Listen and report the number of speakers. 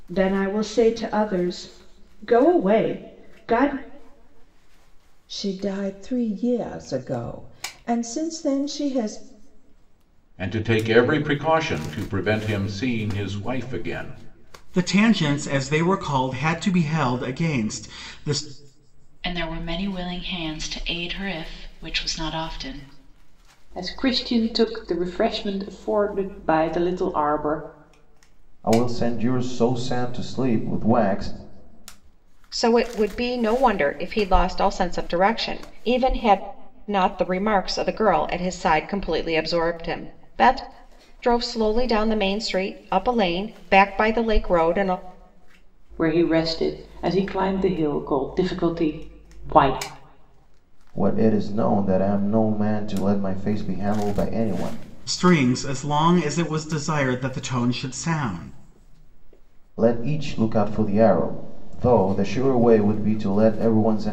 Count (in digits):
8